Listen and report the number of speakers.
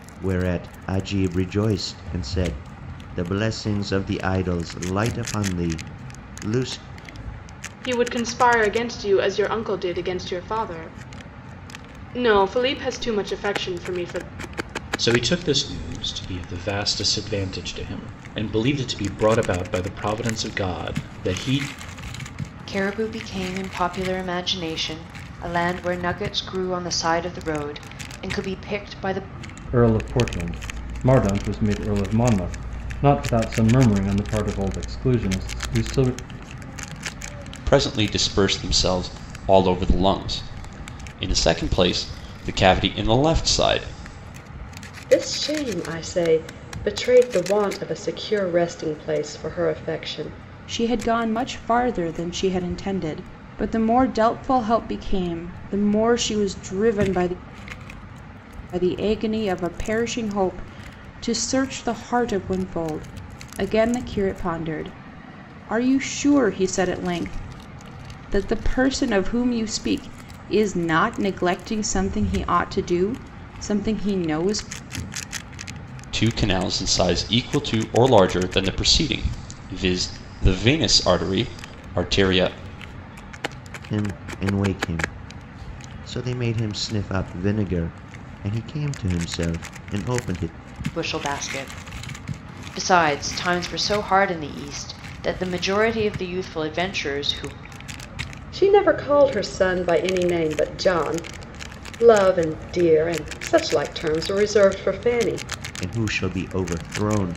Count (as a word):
eight